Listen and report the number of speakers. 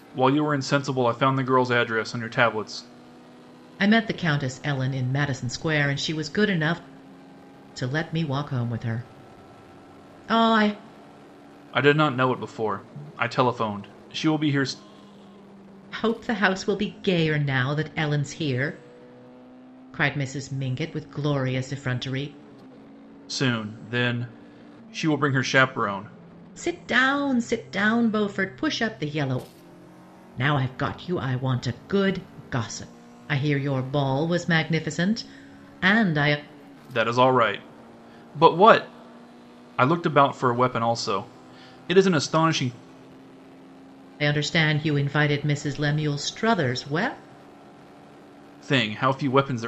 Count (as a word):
two